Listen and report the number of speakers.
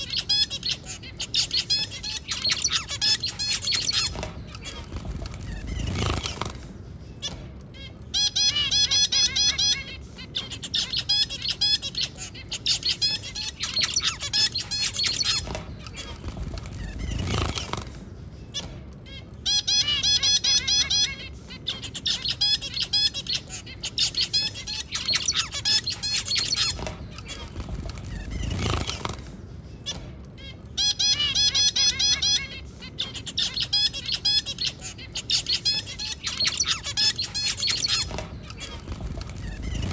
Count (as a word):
zero